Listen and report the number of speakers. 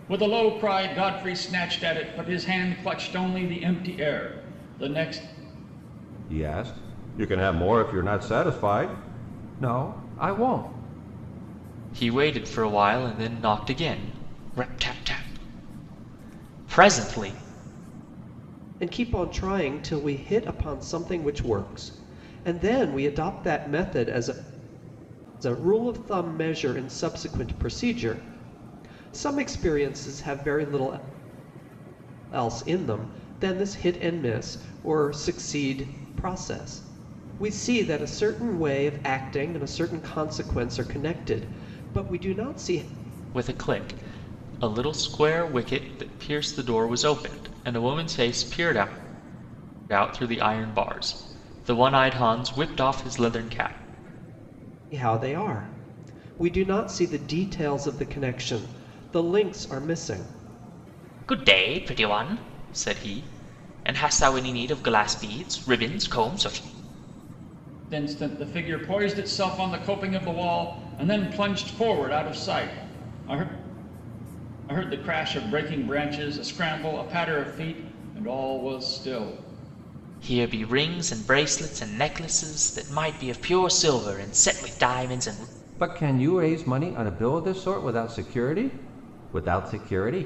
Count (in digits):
4